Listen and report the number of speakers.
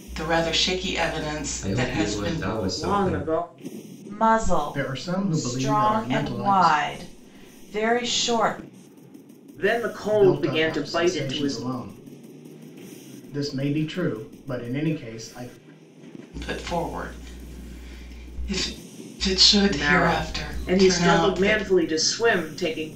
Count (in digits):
5